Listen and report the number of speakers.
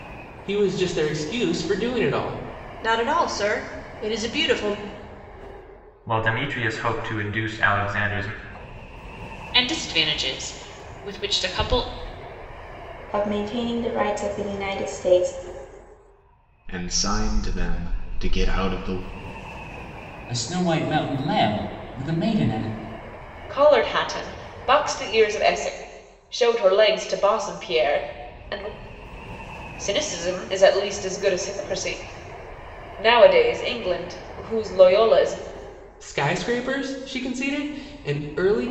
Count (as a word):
eight